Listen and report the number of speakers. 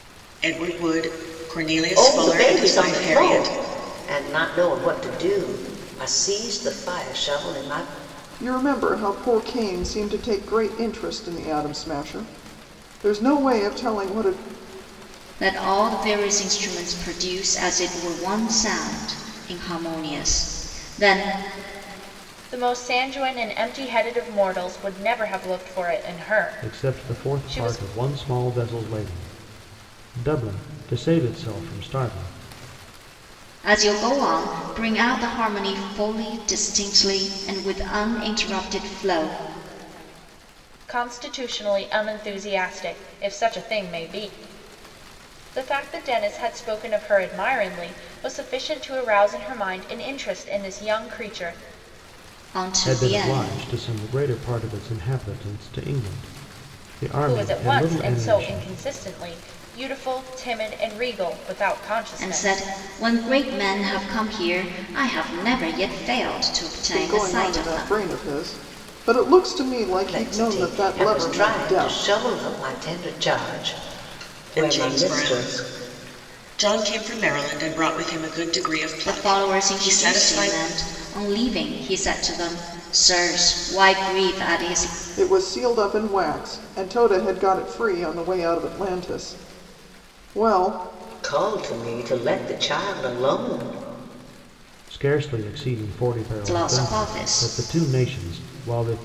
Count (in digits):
6